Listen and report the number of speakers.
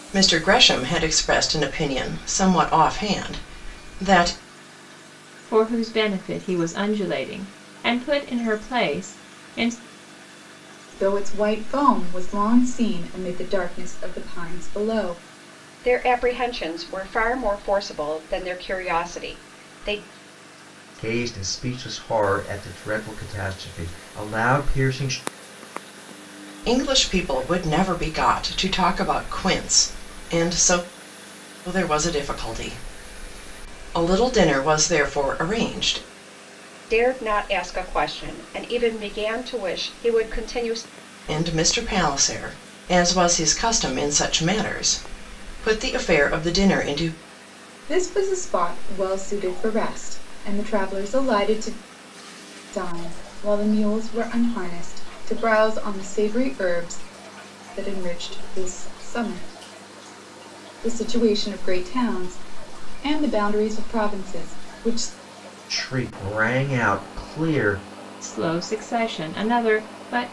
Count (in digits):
5